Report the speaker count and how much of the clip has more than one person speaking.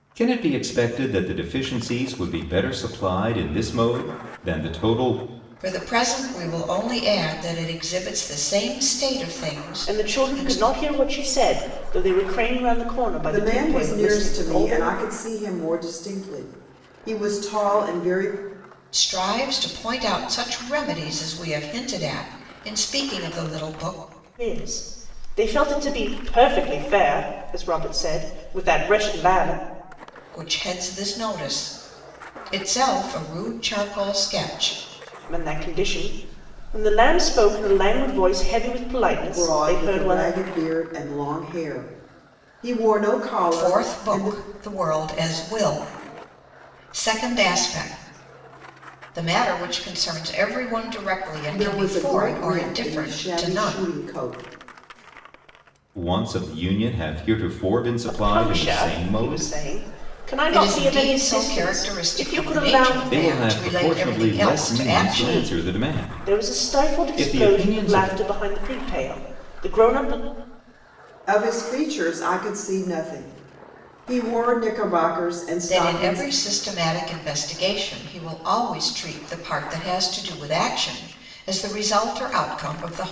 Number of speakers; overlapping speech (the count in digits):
4, about 20%